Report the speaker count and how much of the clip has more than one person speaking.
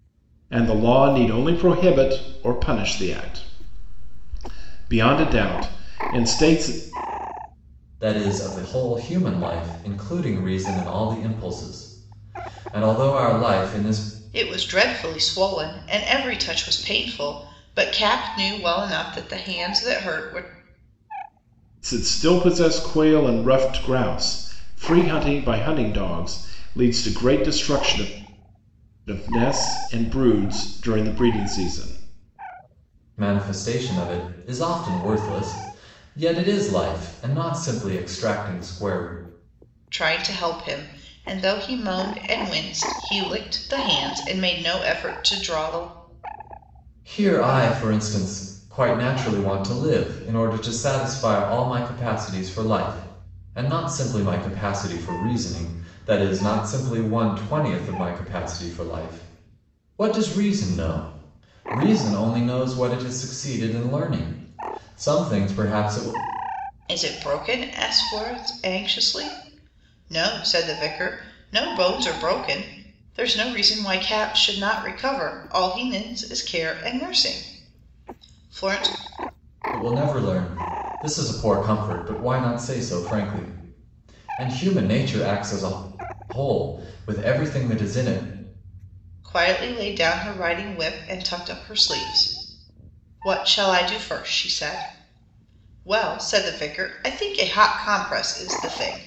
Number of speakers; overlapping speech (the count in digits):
3, no overlap